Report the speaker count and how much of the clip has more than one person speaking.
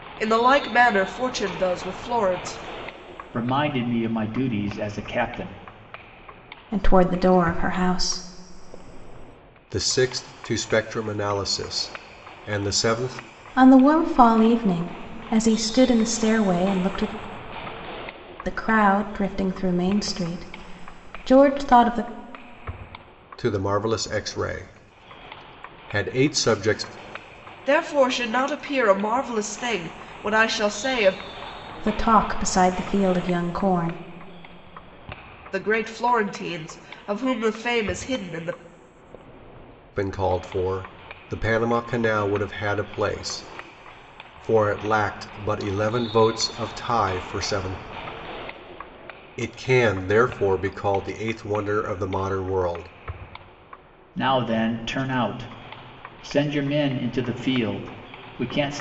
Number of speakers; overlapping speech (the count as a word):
four, no overlap